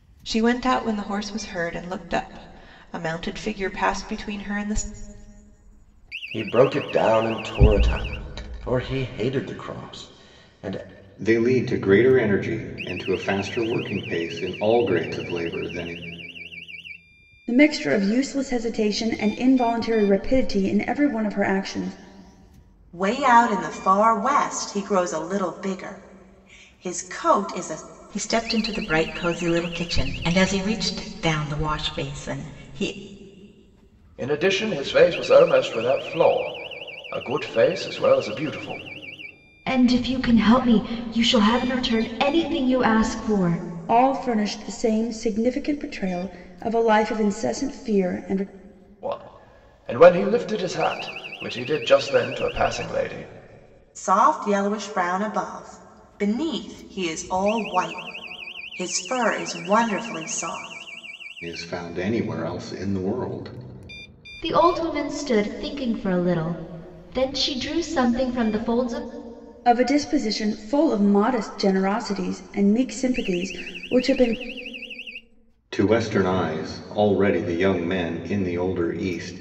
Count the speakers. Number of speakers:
8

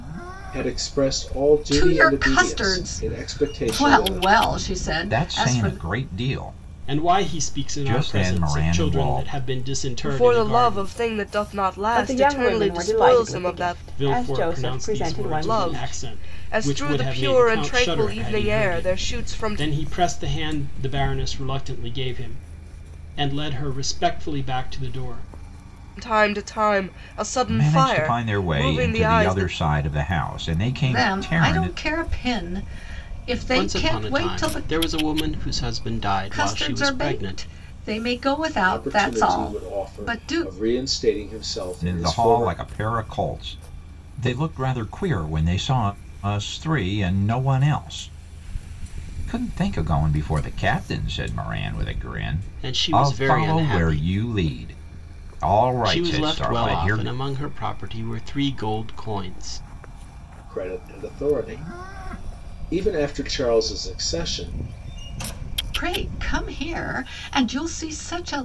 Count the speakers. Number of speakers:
6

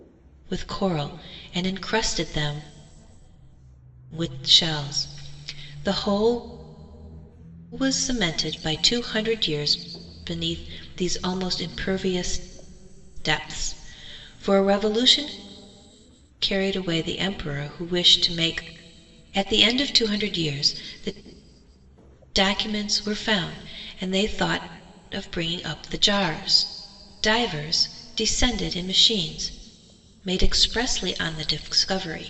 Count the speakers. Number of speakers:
1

